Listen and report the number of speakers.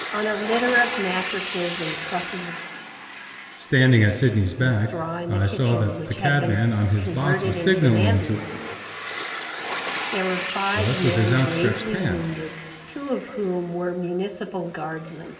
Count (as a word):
two